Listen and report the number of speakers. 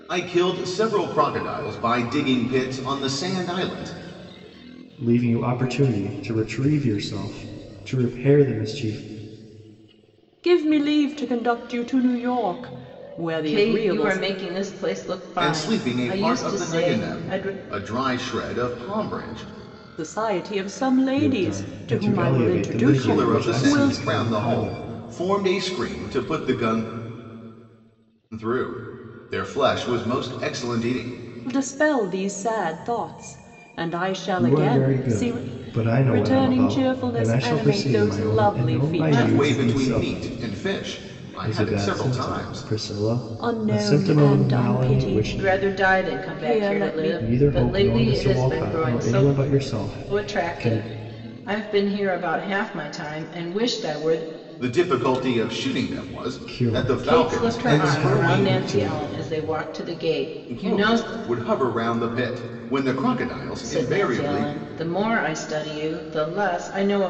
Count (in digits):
4